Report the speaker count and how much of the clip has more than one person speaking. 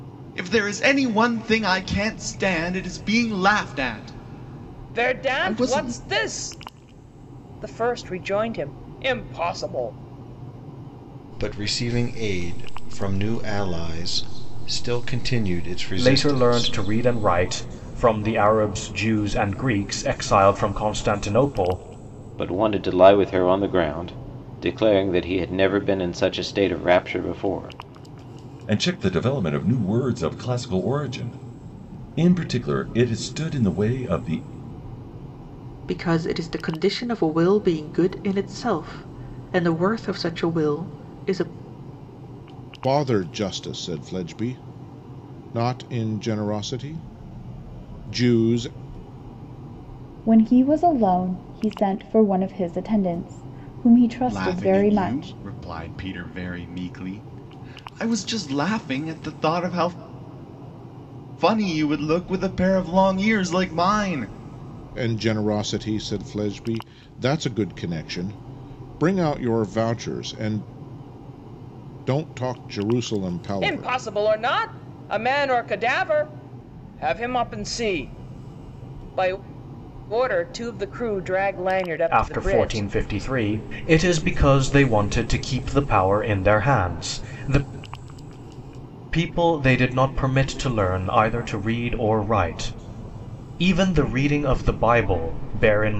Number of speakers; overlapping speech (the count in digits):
9, about 4%